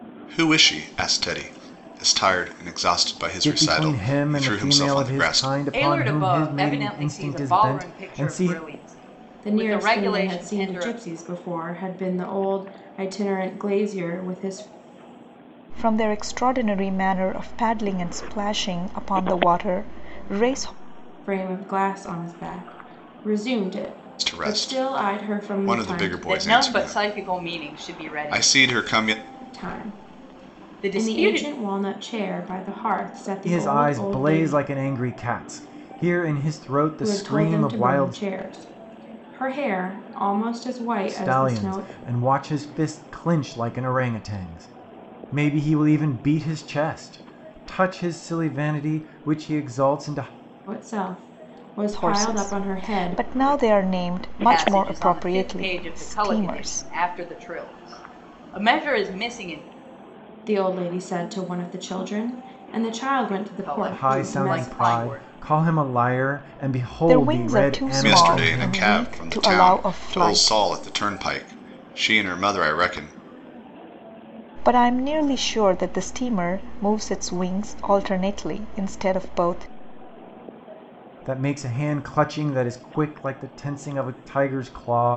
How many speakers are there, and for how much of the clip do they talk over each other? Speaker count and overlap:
5, about 30%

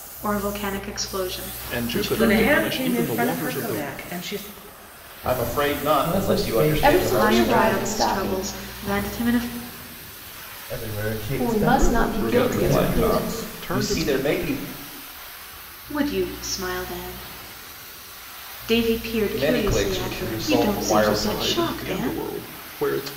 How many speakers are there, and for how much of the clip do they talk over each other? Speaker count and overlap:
6, about 45%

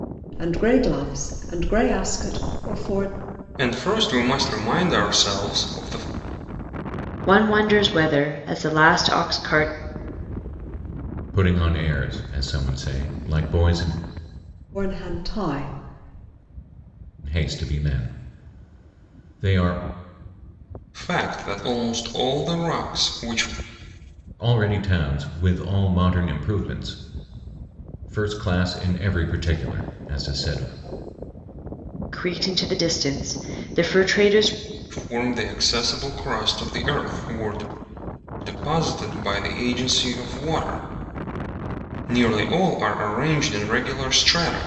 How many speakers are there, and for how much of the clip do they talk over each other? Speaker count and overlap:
4, no overlap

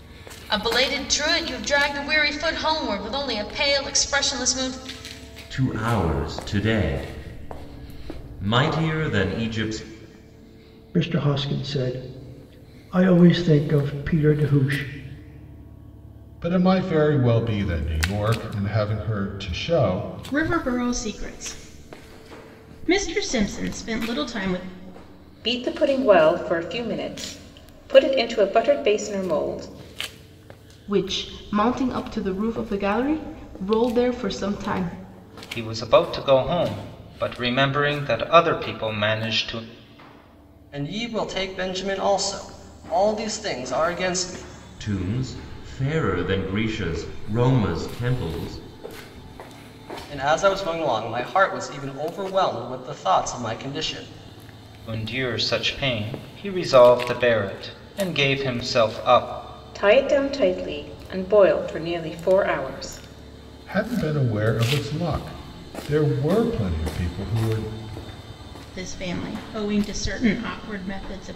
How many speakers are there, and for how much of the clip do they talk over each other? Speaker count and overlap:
9, no overlap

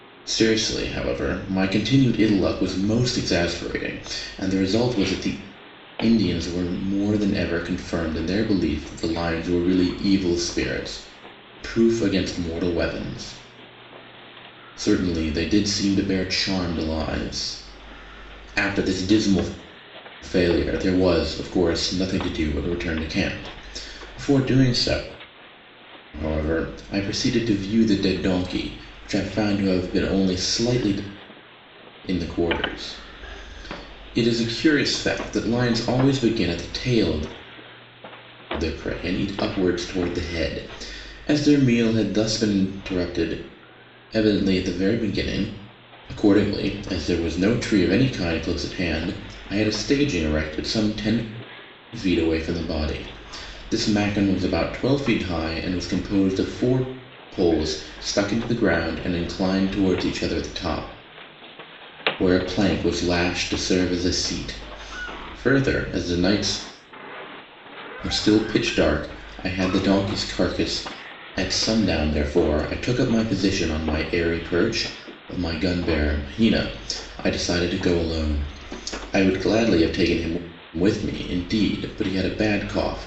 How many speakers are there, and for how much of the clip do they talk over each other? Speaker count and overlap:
1, no overlap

